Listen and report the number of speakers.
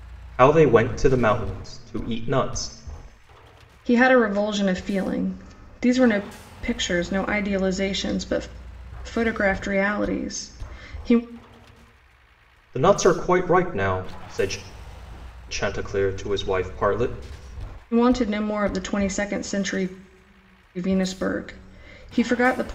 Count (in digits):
2